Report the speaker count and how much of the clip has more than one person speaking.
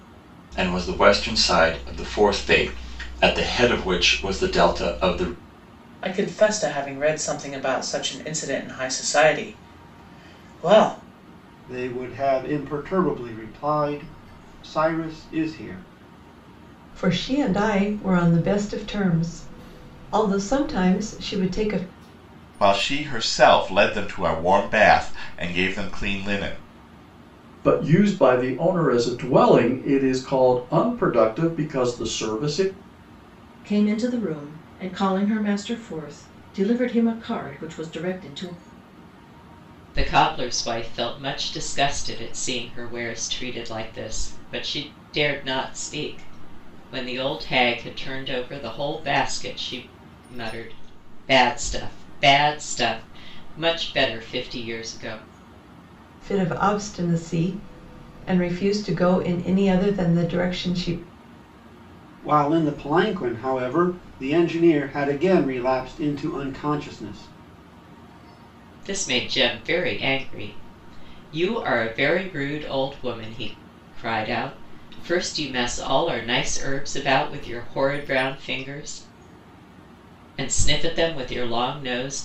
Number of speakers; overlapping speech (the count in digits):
8, no overlap